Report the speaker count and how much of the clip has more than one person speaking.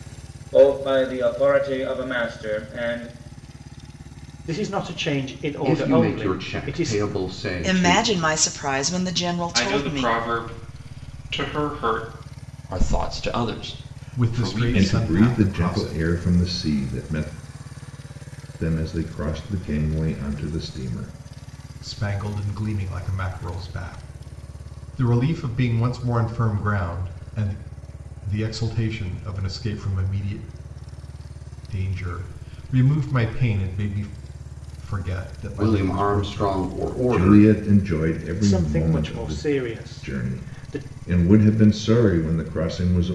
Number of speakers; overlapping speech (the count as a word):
eight, about 18%